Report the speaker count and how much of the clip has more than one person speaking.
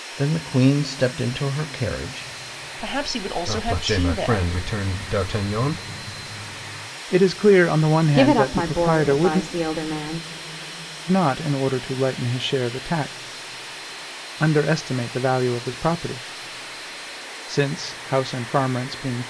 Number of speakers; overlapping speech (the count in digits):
5, about 12%